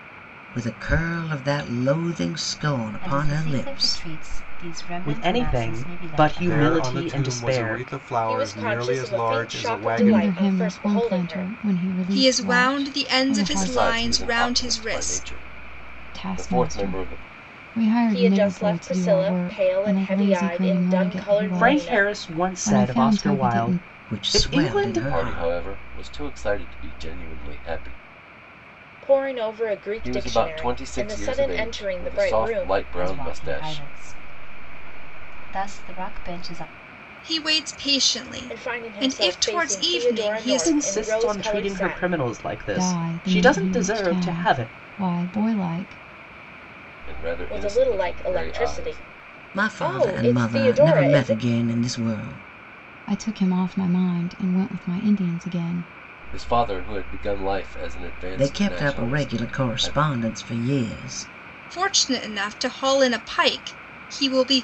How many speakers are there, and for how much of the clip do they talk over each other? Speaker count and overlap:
eight, about 52%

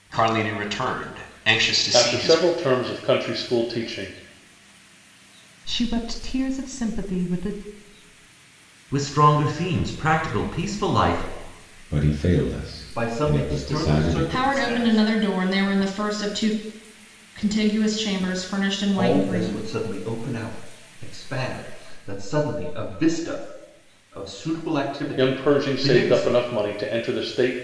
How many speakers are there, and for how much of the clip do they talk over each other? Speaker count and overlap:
seven, about 17%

